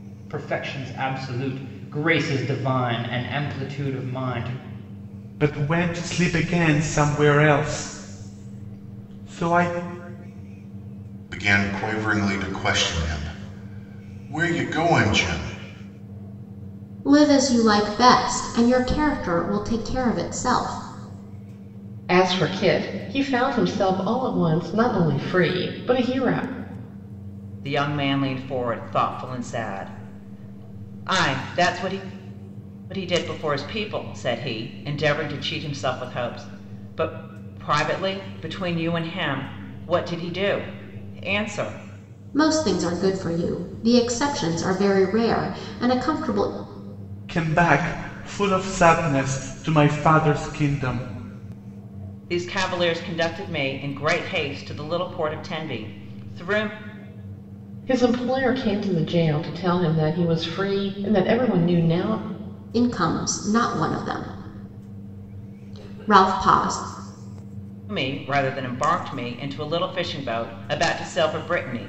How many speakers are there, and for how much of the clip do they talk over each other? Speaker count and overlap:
six, no overlap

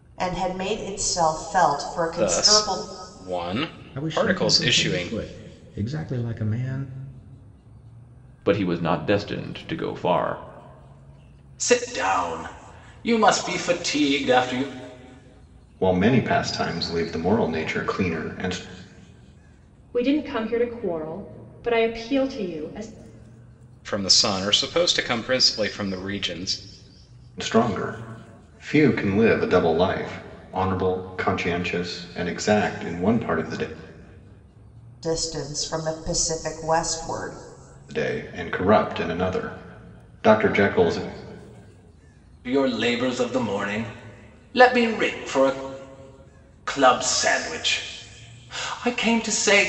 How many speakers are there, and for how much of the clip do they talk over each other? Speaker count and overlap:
seven, about 4%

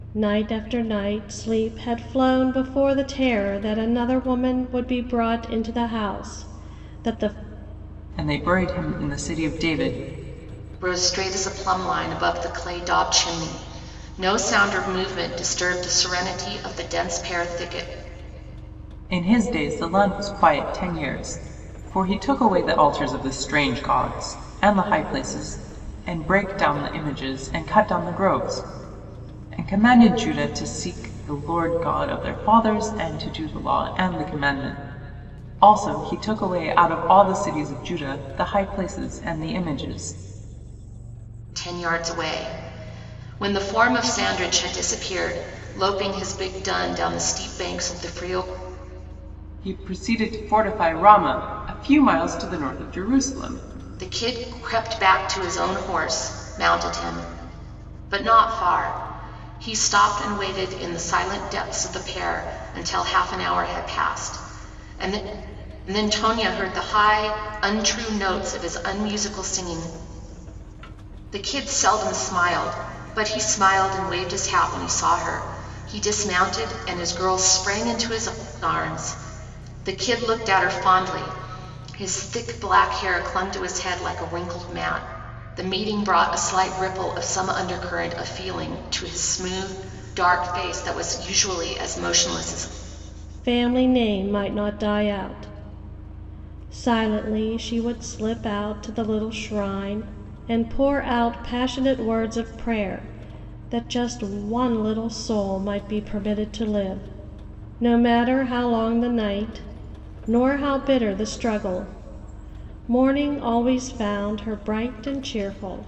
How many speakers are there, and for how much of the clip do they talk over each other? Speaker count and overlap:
three, no overlap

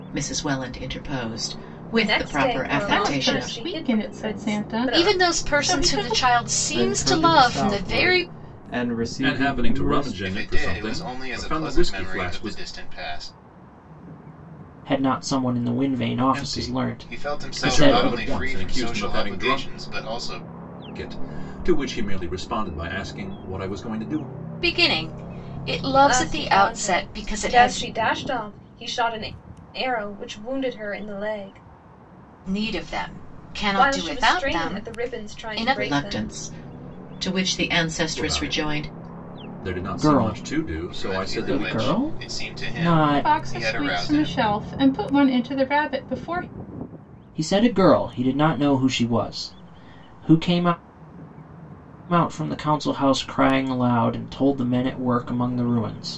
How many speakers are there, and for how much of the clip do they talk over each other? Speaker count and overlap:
eight, about 40%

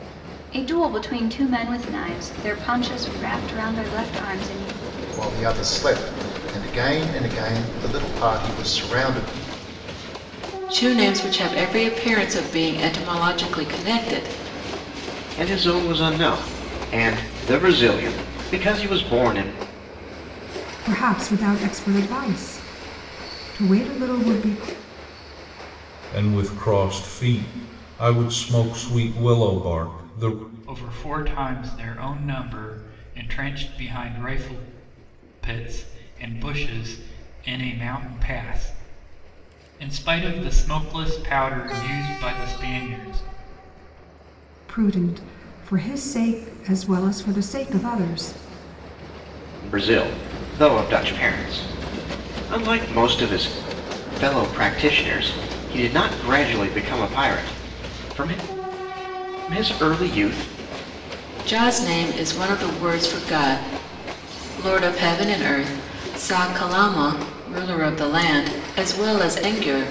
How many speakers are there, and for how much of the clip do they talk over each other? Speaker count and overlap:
seven, no overlap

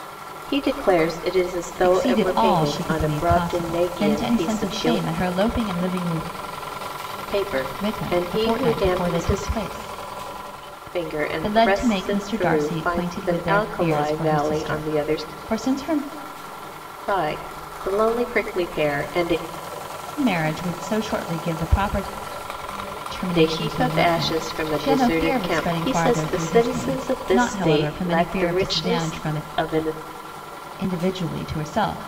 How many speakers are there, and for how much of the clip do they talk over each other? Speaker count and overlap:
two, about 46%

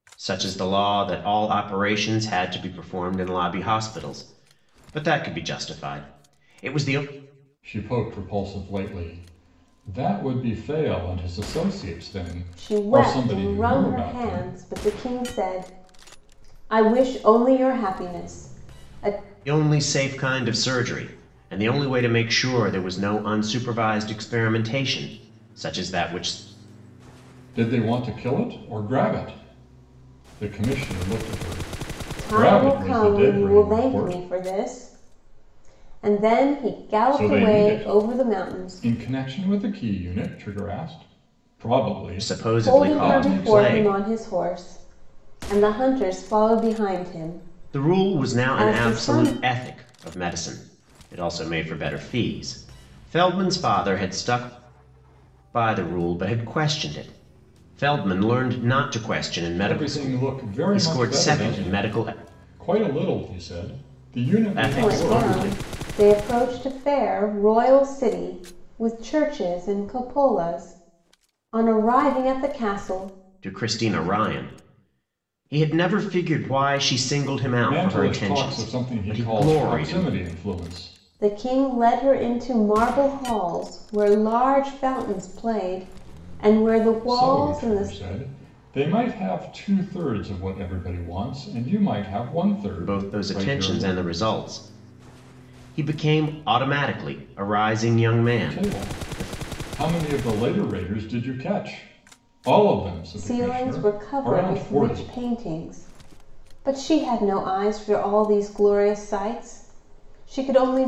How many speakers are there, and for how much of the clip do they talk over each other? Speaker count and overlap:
three, about 18%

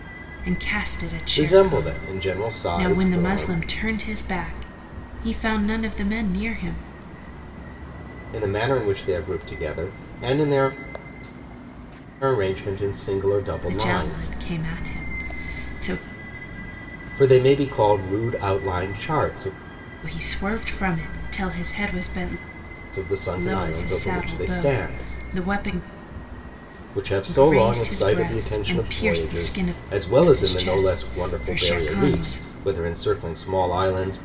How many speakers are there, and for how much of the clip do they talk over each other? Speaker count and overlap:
two, about 26%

